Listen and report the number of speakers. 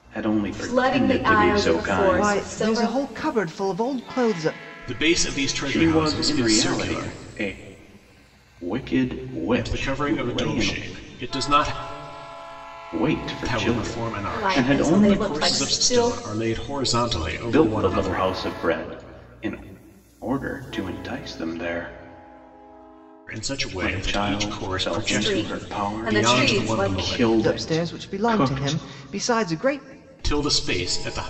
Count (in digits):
4